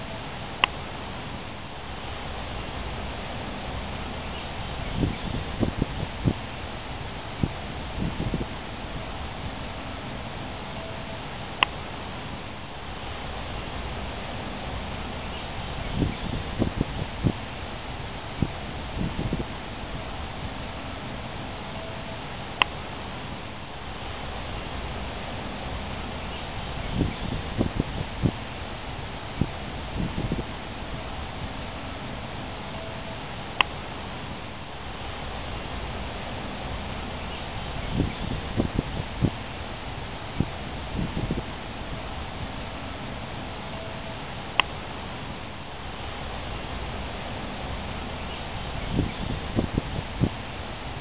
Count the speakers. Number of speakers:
0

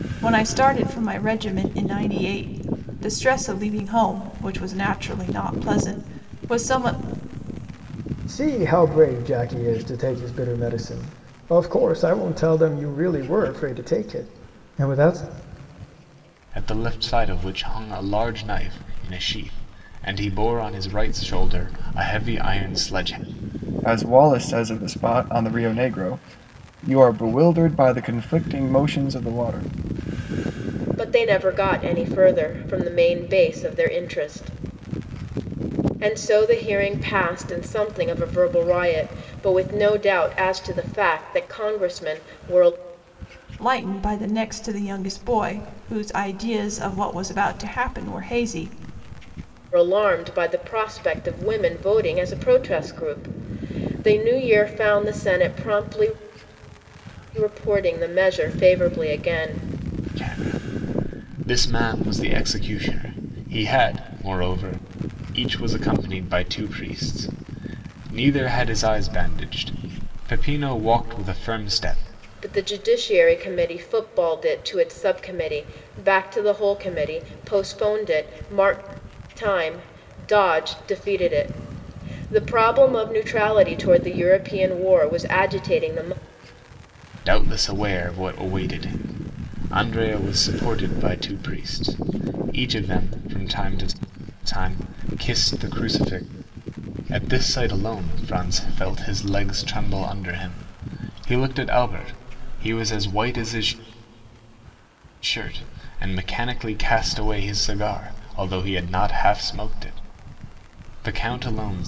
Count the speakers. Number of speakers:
5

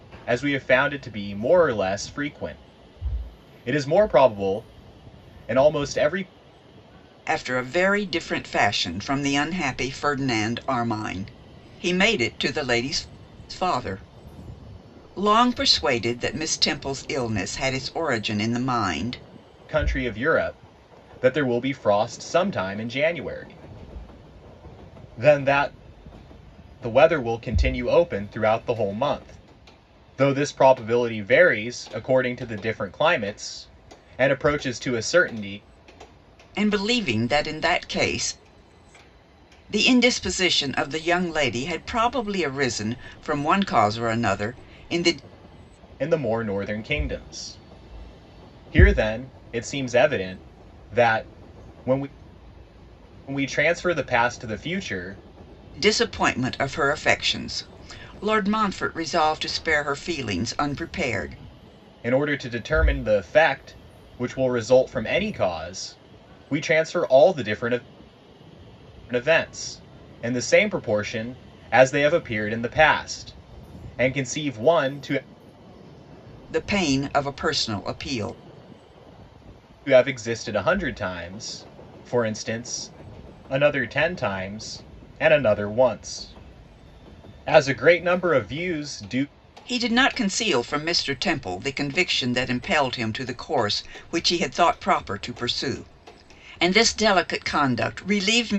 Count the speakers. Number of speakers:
2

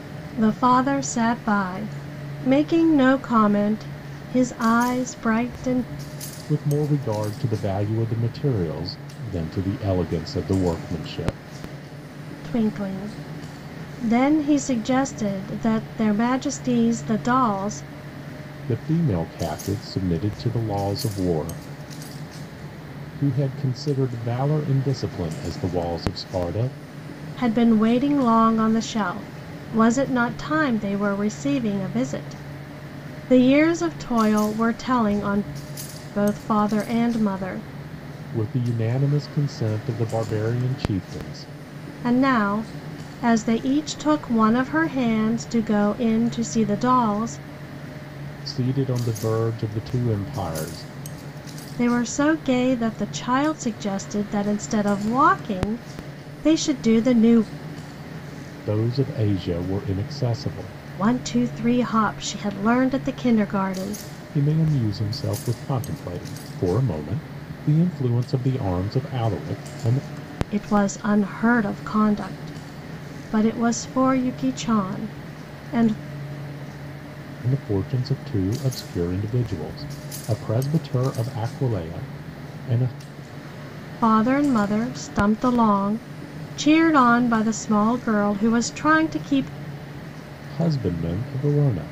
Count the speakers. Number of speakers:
2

